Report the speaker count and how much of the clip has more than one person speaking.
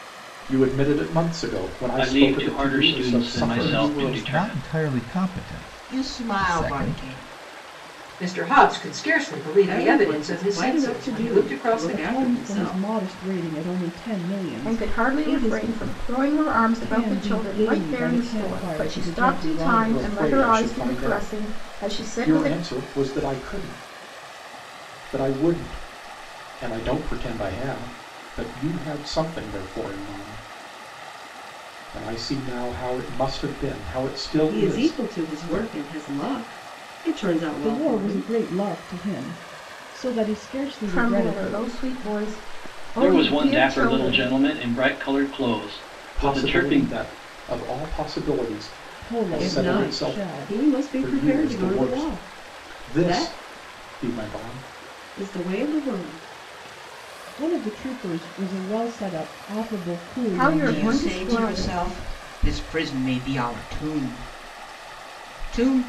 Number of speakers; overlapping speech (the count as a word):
eight, about 37%